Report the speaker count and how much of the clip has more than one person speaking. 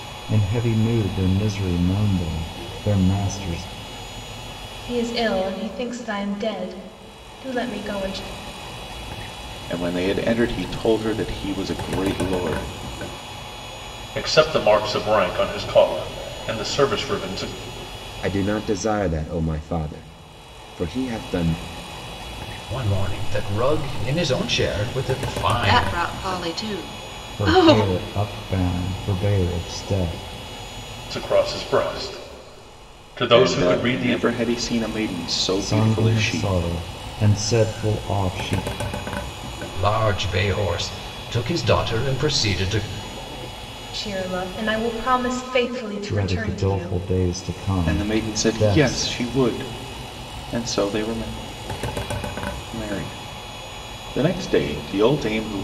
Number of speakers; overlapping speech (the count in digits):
7, about 9%